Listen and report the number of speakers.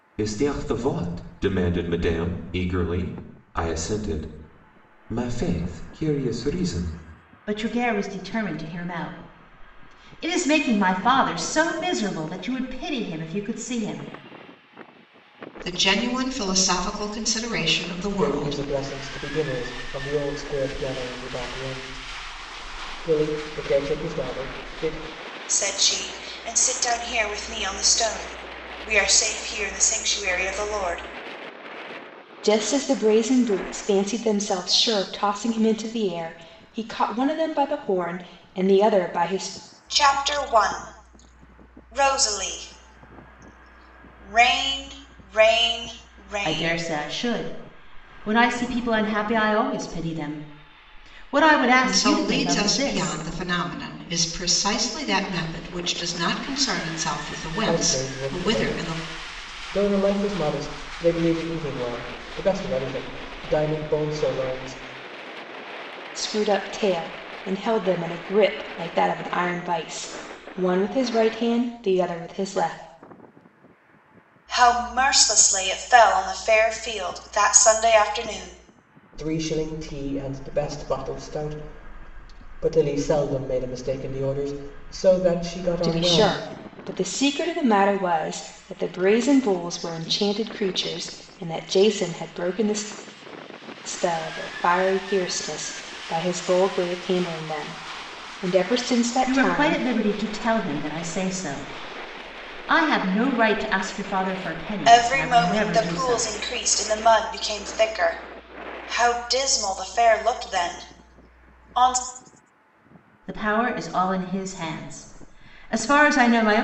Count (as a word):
six